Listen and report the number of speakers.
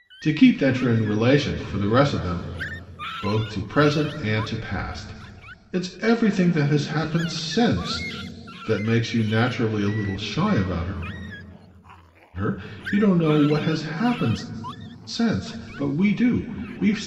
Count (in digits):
1